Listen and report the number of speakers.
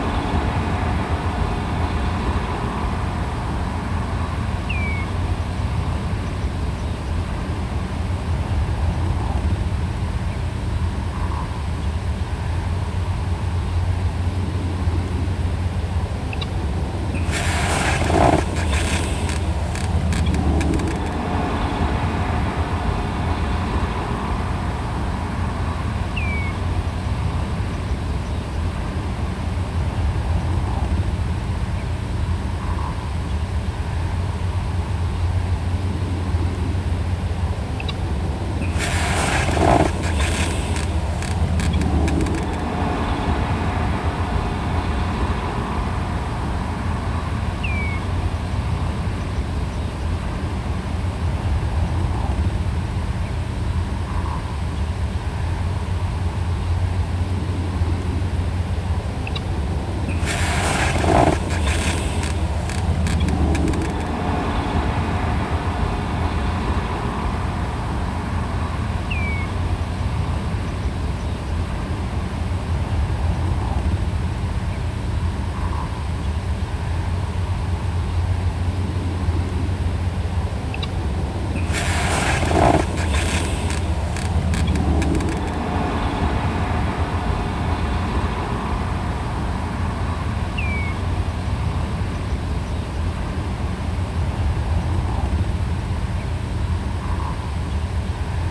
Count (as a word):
zero